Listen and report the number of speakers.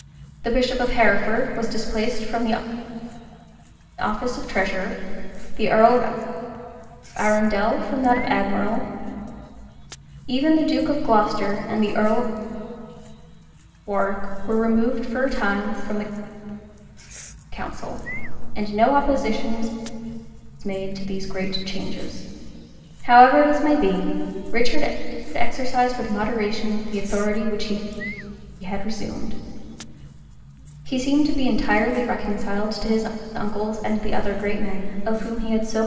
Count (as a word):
one